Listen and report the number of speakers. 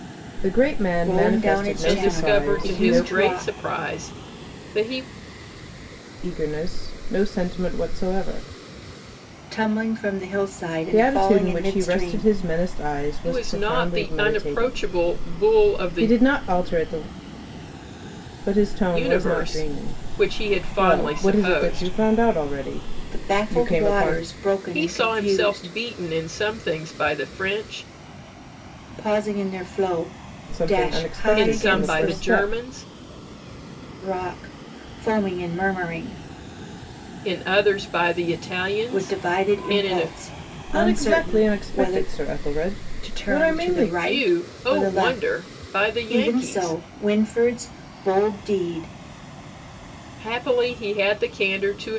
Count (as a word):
three